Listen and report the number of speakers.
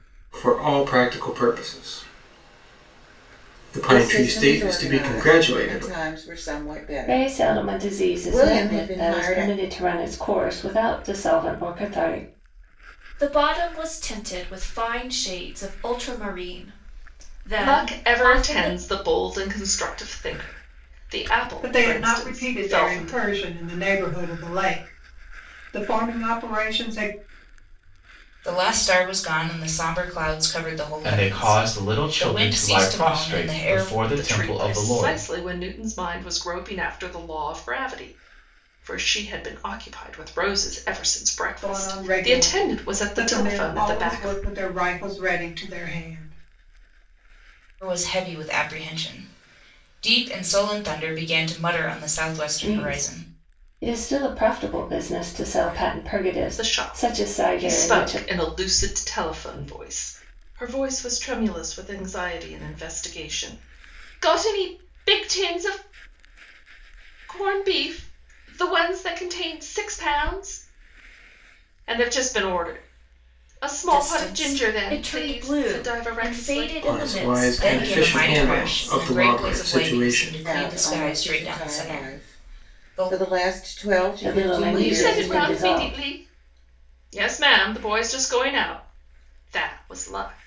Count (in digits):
8